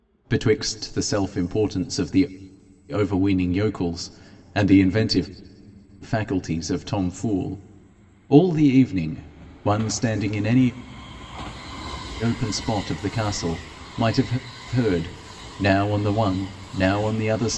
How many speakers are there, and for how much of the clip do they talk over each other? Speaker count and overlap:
one, no overlap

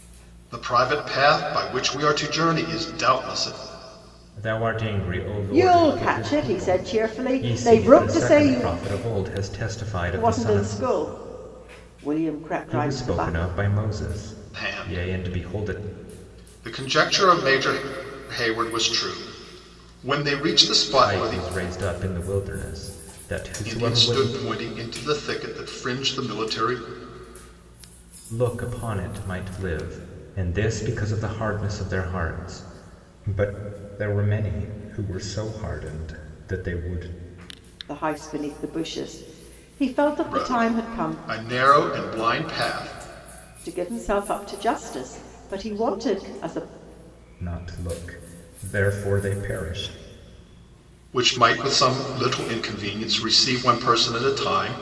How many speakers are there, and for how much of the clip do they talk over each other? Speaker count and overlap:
three, about 14%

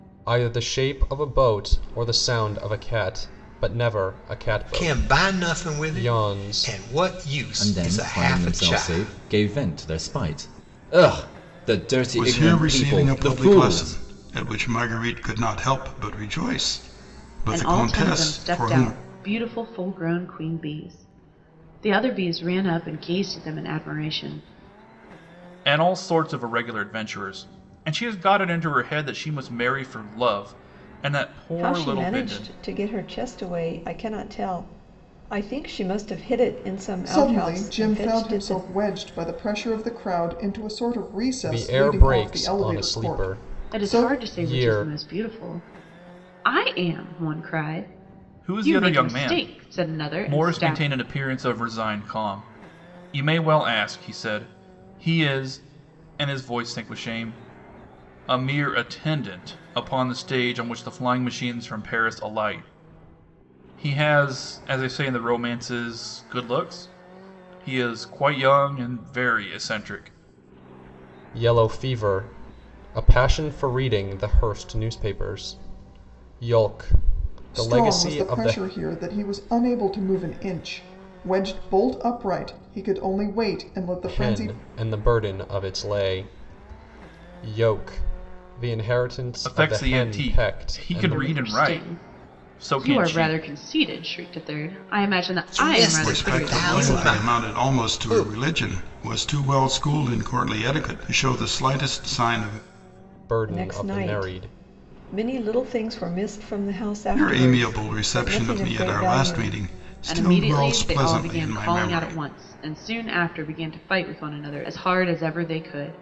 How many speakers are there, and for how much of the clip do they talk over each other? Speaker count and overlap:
eight, about 26%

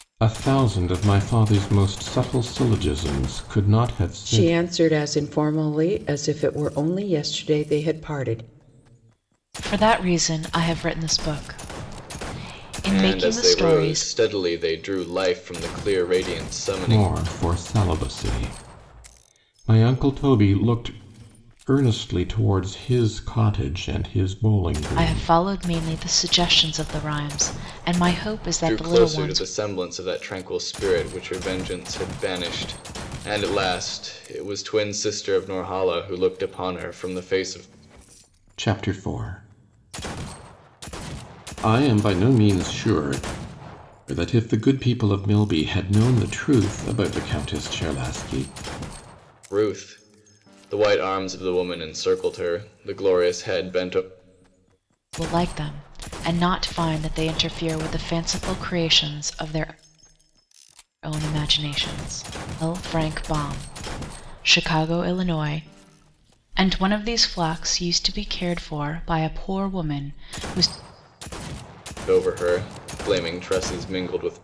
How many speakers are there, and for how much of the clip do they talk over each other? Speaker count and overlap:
four, about 4%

